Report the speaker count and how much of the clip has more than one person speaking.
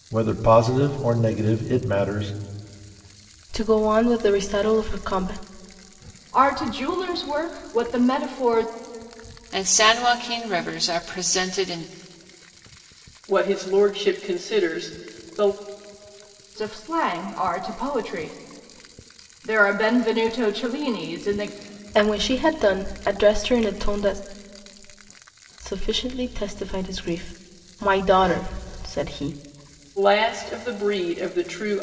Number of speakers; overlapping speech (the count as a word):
five, no overlap